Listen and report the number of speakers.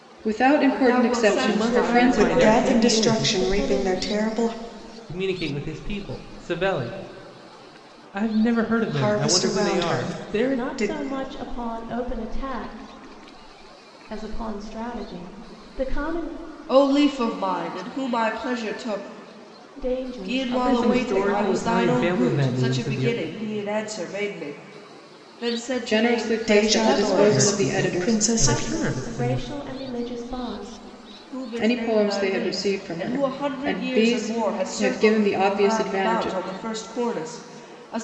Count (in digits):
5